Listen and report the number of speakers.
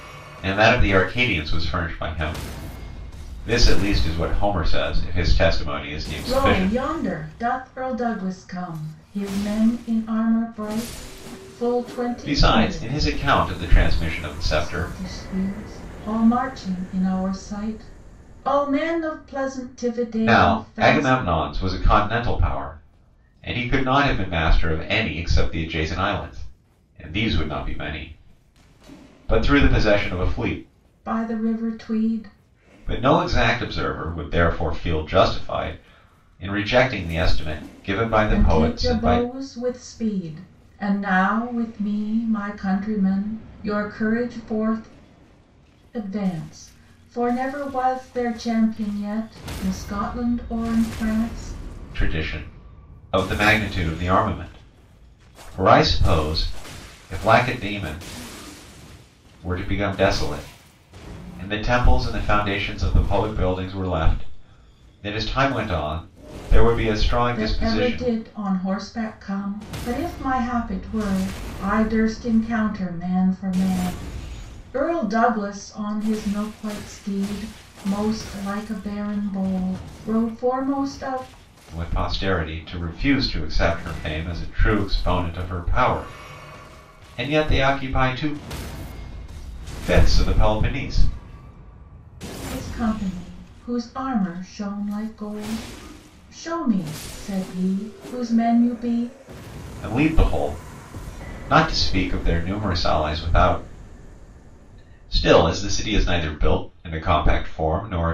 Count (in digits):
2